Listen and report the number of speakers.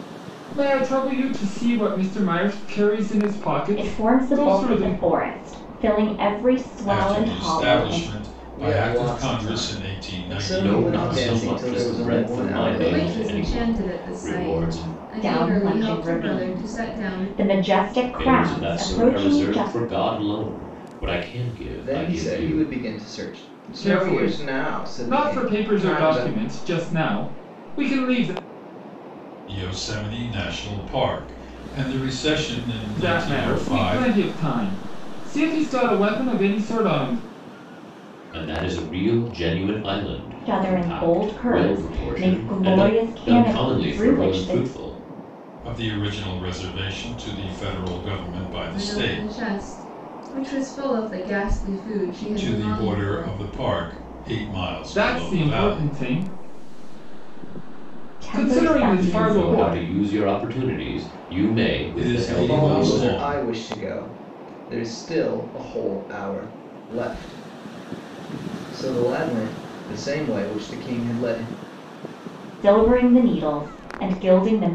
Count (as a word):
six